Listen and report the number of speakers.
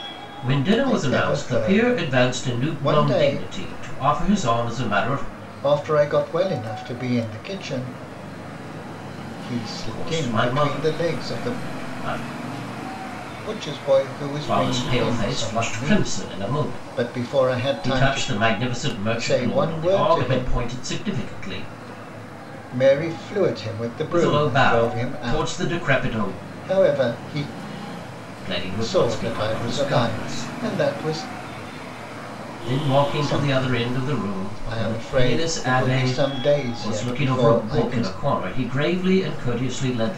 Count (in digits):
2